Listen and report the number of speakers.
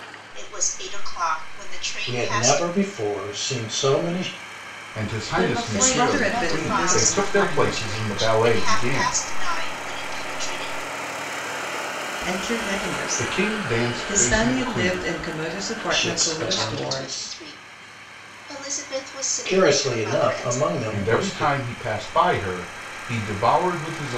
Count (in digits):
5